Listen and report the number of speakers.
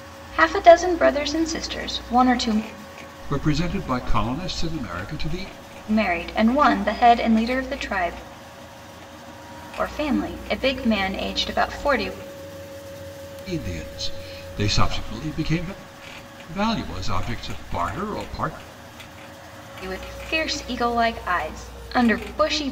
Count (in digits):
2